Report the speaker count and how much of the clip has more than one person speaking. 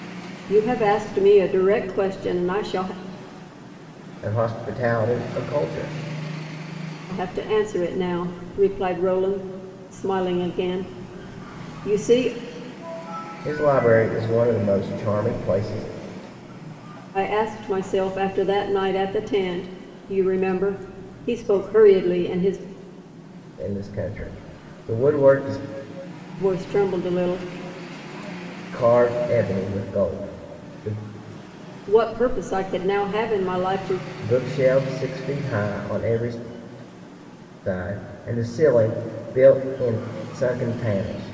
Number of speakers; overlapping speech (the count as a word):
two, no overlap